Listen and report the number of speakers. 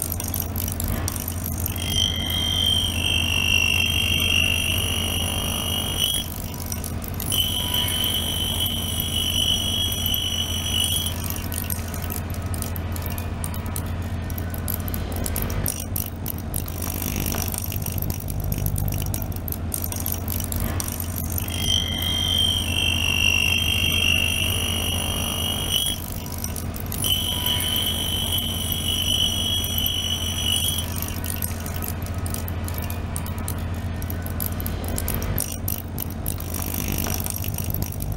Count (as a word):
zero